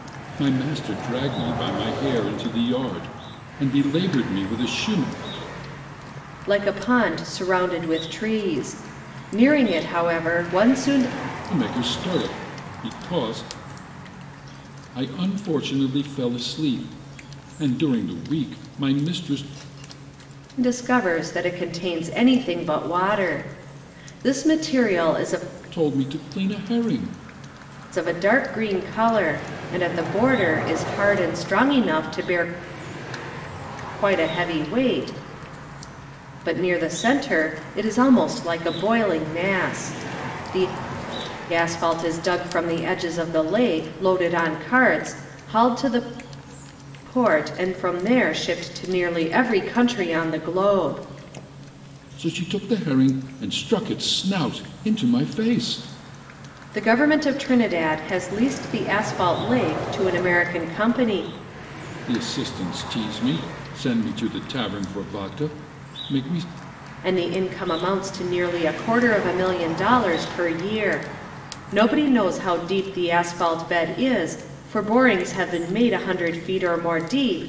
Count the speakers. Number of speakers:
two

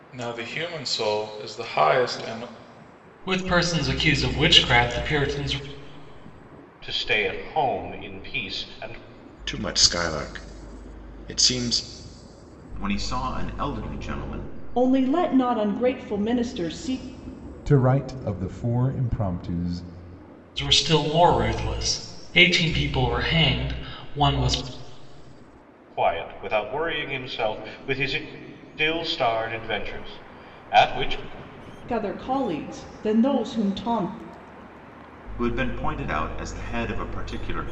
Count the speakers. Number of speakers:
seven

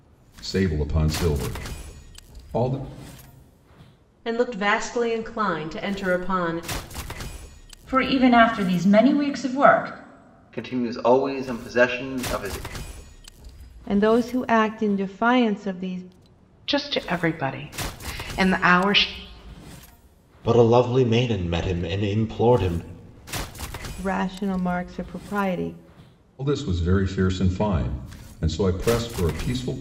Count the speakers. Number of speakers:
seven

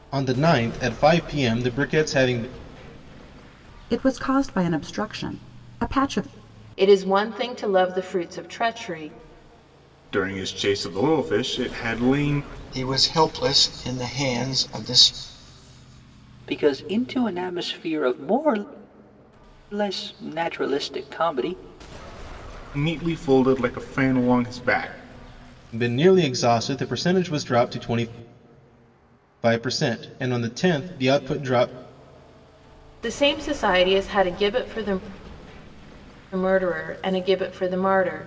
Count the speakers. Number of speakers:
six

